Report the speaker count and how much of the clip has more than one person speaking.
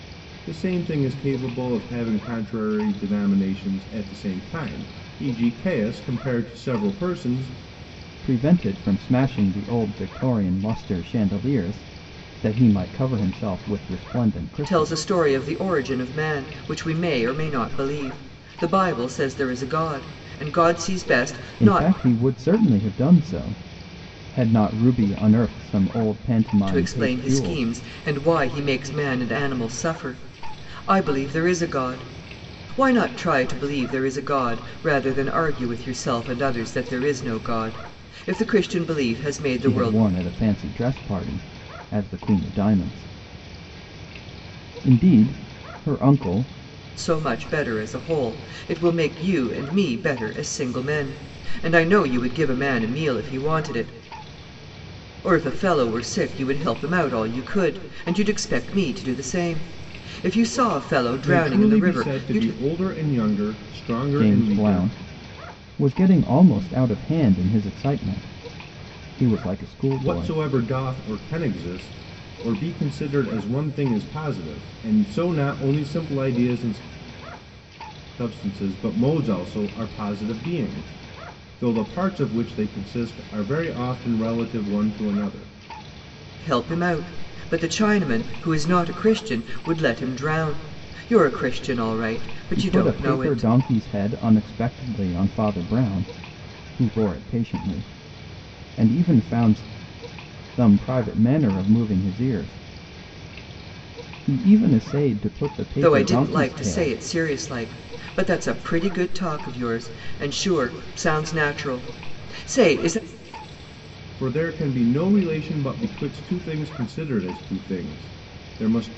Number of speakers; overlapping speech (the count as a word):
three, about 6%